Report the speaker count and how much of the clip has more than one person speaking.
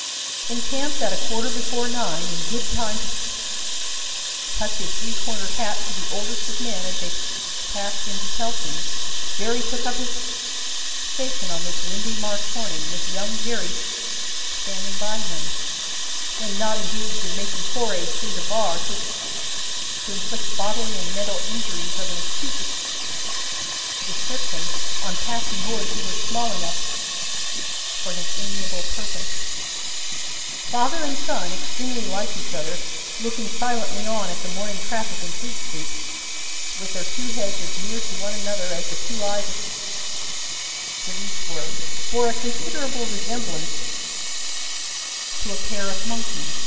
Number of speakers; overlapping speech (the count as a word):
one, no overlap